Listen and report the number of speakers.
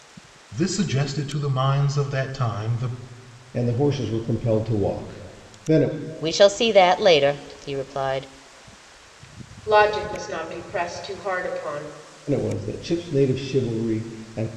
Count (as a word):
four